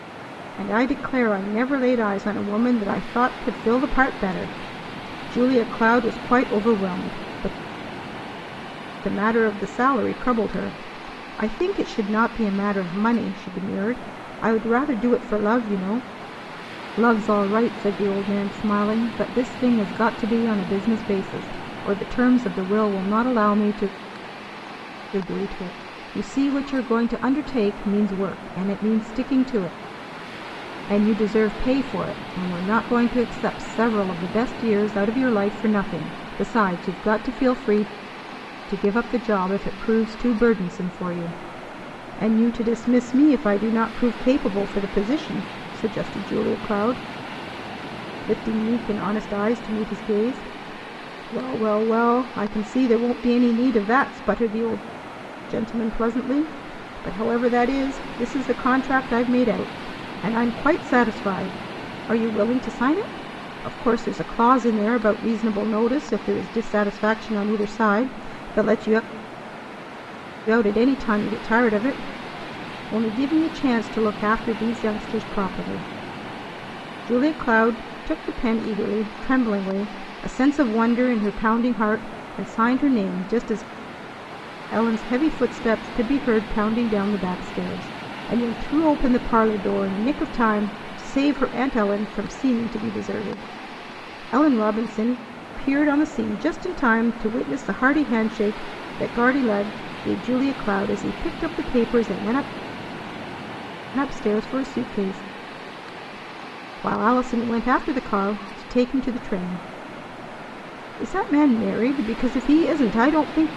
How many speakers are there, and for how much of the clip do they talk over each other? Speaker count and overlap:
one, no overlap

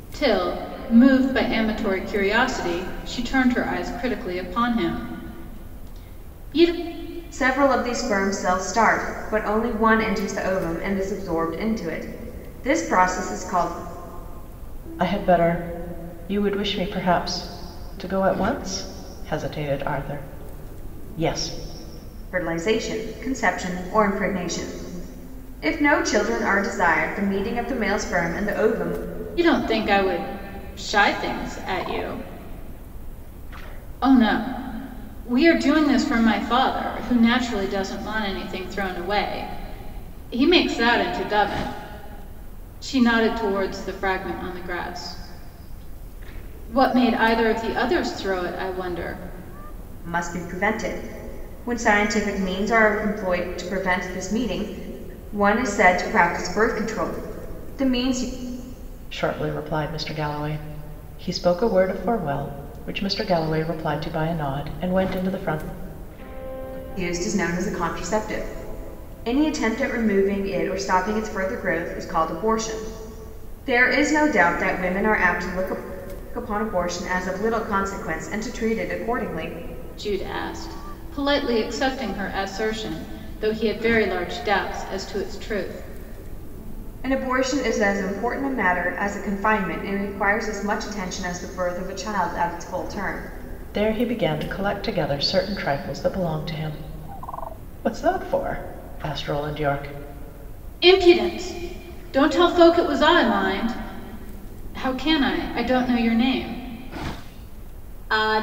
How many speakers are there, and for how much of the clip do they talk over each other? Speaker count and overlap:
three, no overlap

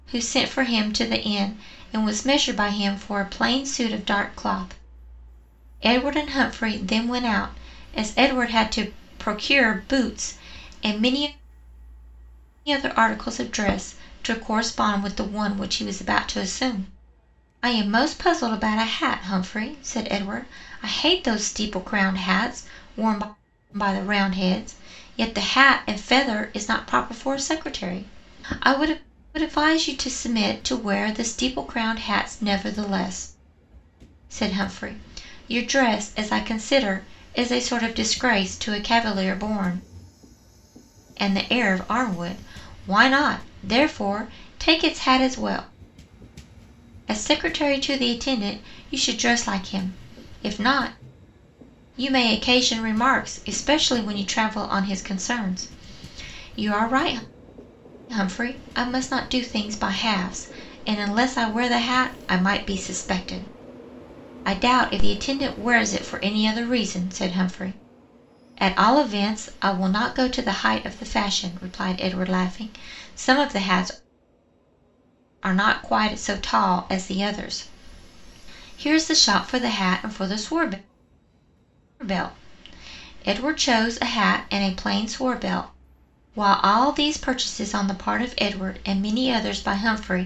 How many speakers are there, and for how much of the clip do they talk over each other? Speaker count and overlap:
one, no overlap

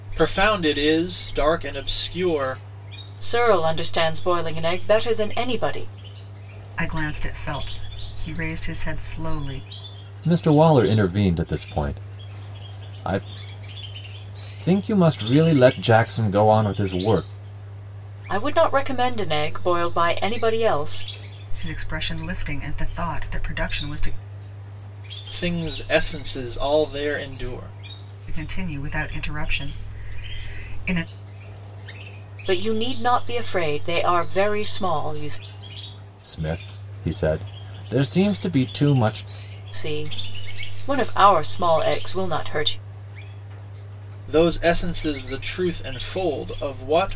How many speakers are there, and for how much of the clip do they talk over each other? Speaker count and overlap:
four, no overlap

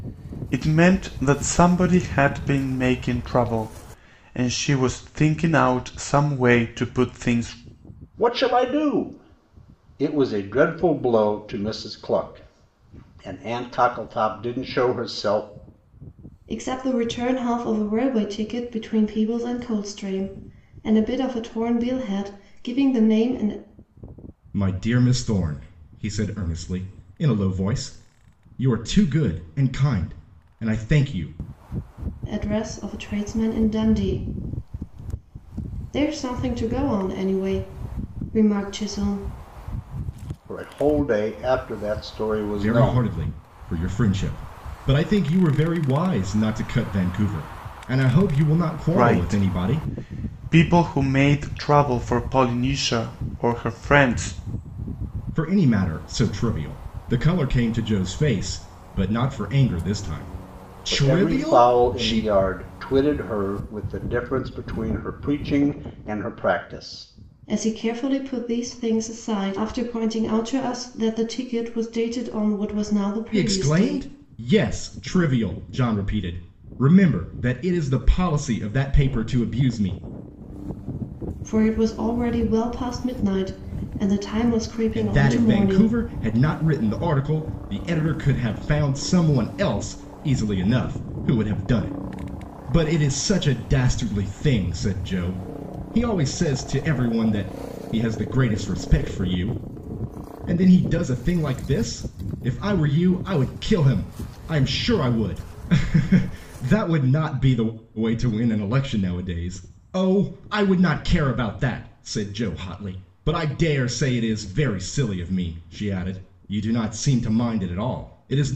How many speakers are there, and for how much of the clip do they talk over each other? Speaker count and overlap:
four, about 4%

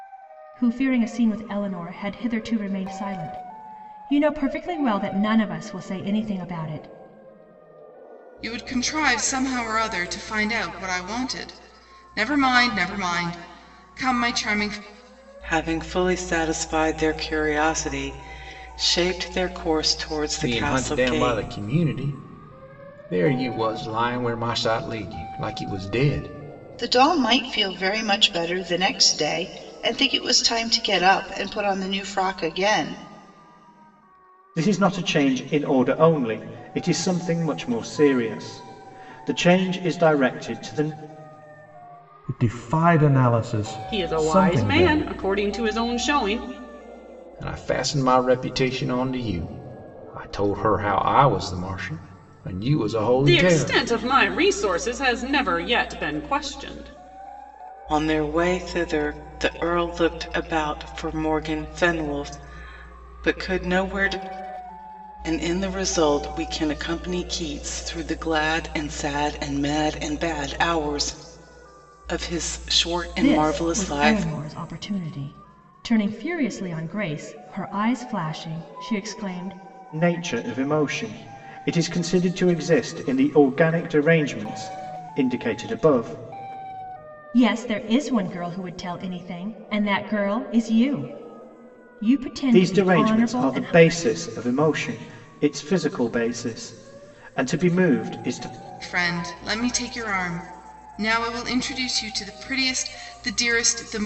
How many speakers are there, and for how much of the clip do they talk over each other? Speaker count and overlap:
eight, about 5%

